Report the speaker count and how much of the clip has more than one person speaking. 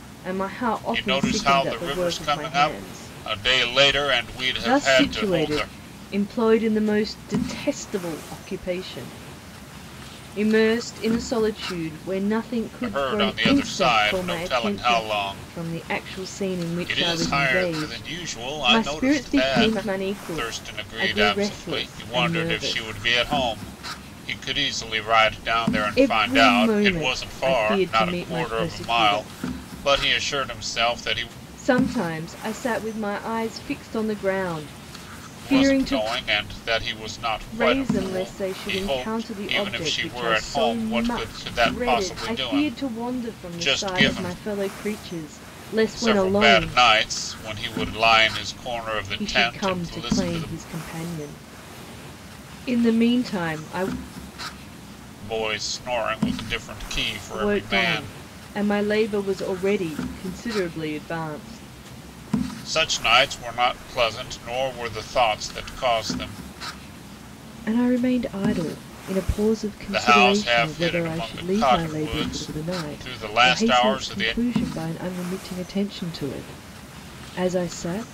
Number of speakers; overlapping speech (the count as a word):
two, about 40%